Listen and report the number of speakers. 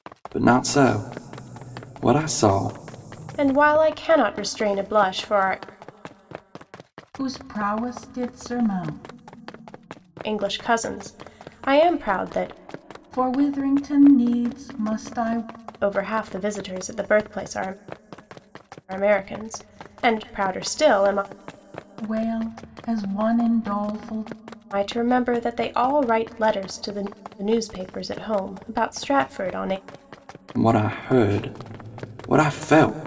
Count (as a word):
three